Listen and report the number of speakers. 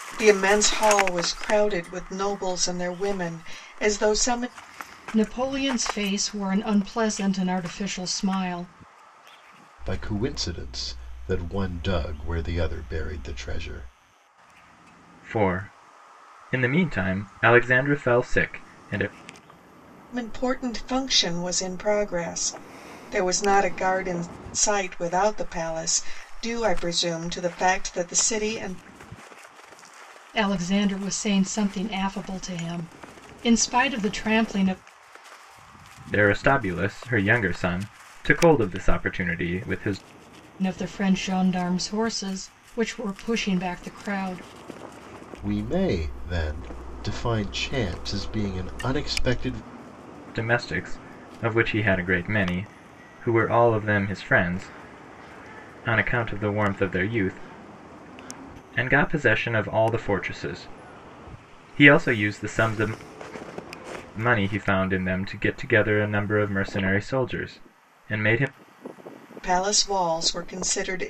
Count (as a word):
four